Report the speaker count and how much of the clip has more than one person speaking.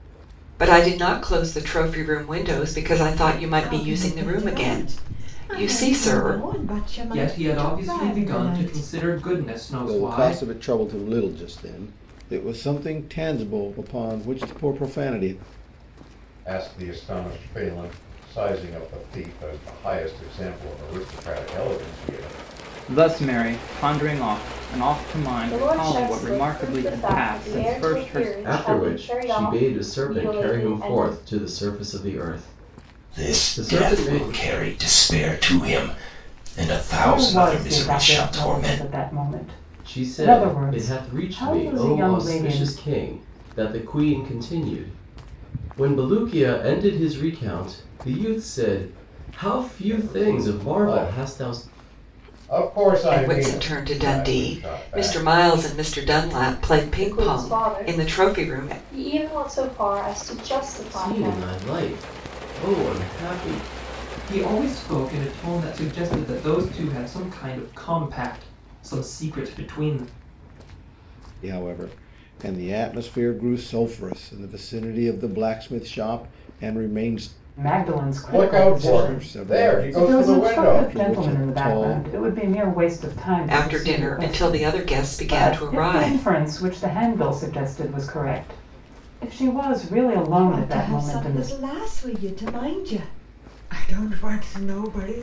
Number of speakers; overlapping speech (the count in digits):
10, about 33%